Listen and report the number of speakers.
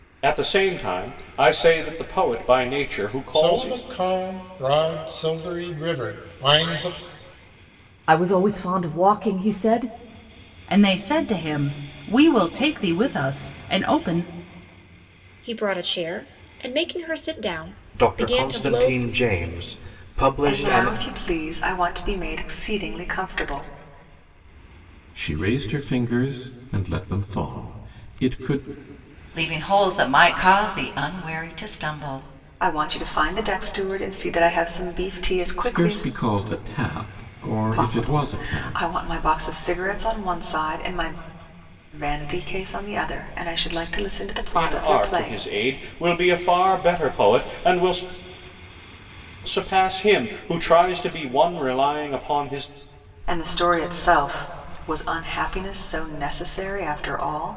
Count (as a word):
nine